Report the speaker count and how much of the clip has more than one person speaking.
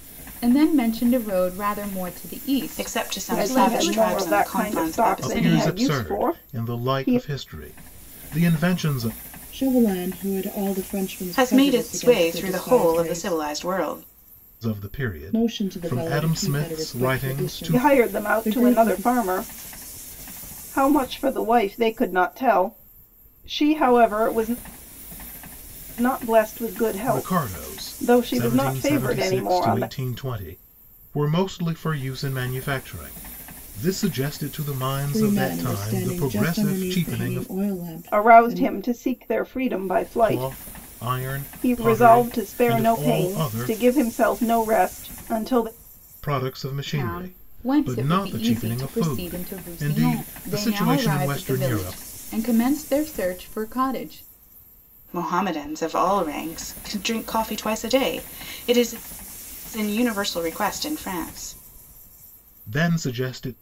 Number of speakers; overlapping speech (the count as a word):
five, about 39%